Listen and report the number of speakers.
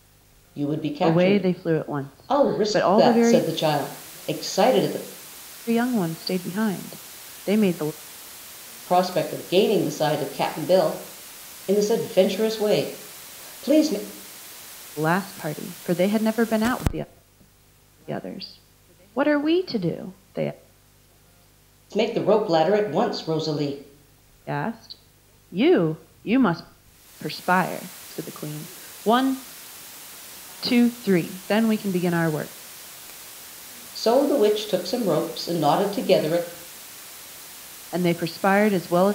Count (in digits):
2